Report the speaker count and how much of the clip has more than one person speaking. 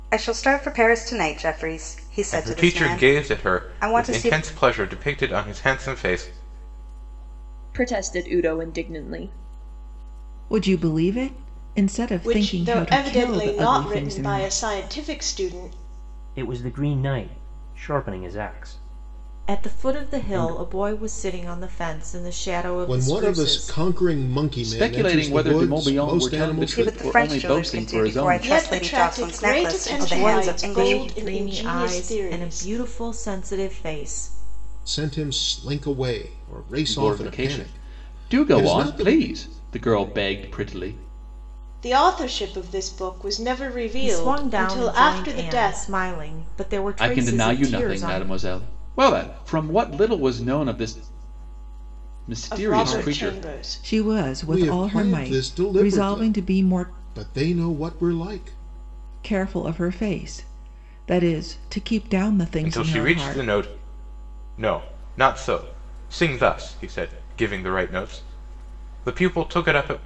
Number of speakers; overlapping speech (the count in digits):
9, about 36%